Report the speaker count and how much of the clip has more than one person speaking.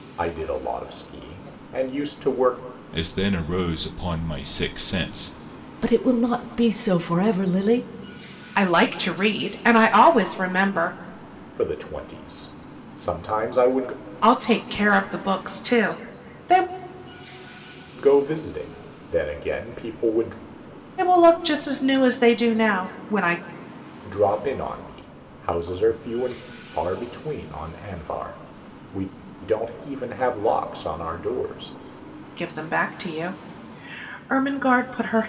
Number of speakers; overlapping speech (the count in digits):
4, no overlap